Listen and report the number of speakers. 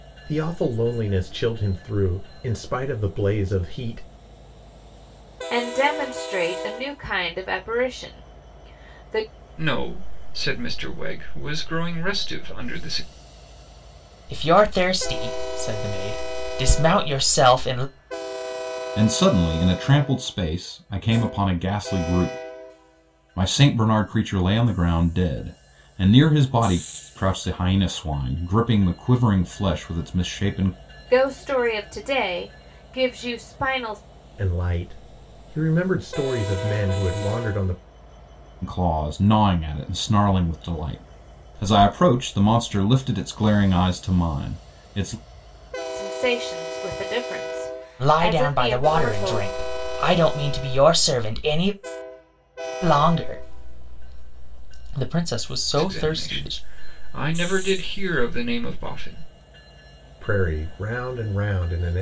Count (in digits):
5